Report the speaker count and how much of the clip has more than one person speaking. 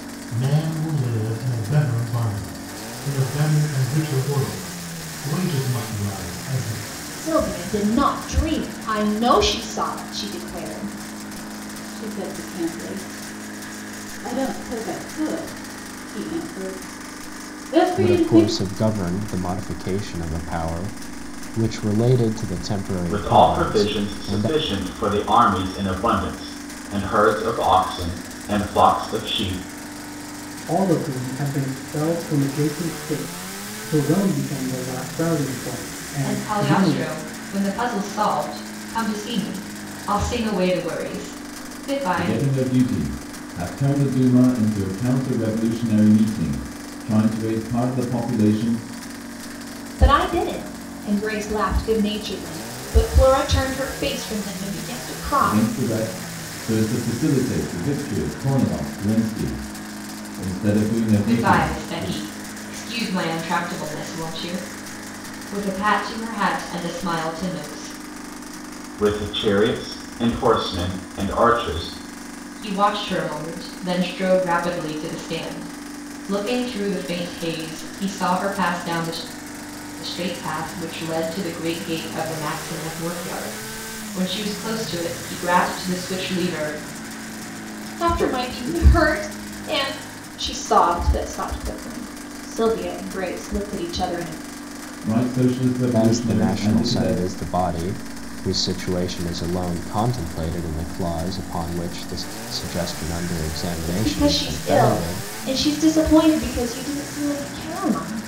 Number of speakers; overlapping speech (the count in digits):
8, about 7%